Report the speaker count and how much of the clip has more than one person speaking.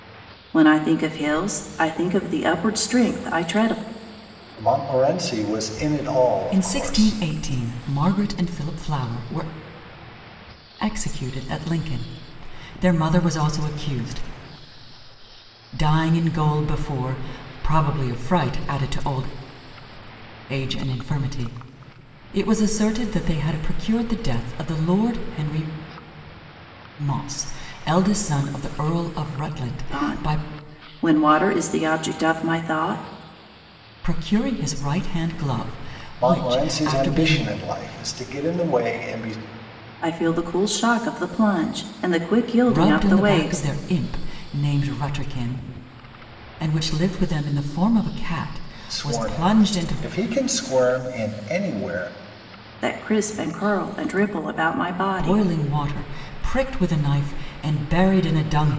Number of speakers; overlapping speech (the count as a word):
three, about 9%